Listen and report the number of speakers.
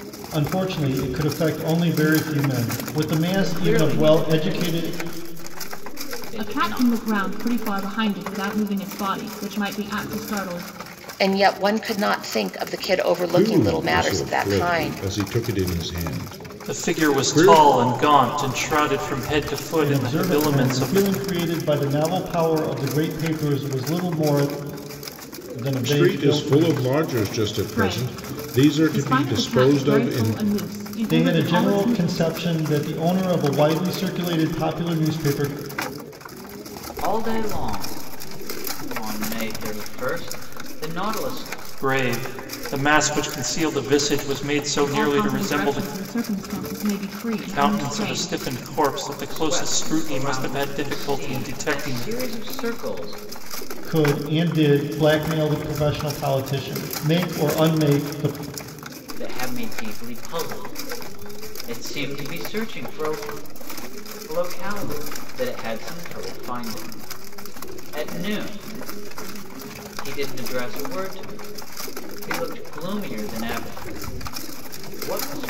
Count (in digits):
6